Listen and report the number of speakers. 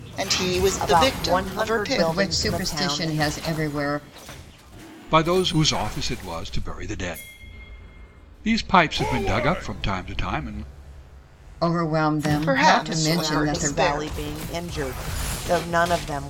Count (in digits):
4